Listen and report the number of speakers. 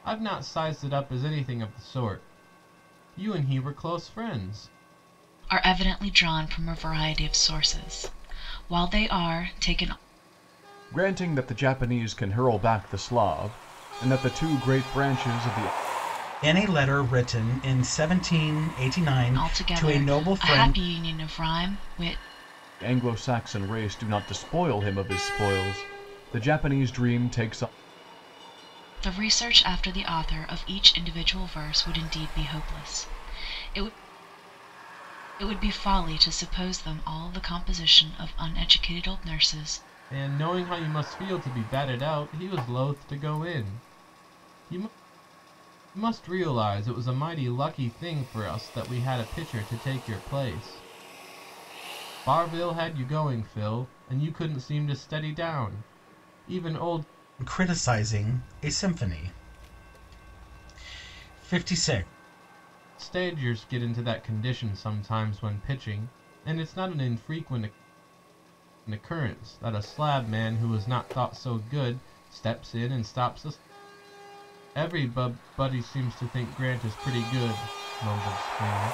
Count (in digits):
4